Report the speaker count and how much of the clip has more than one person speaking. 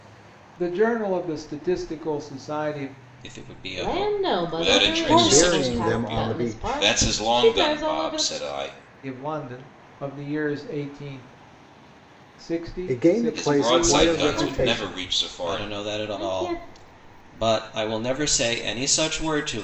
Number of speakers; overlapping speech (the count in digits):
5, about 43%